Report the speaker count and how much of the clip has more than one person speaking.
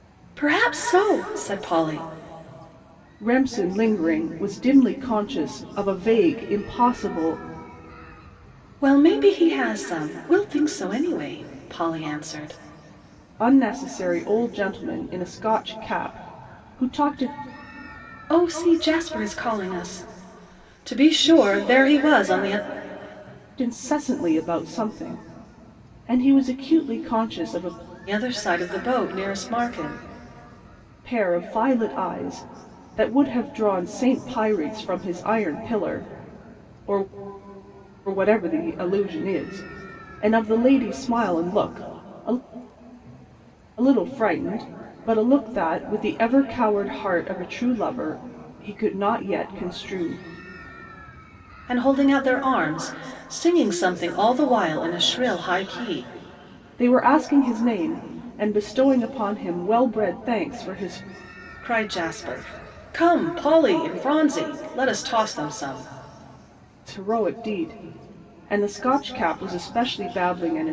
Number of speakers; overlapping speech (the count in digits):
2, no overlap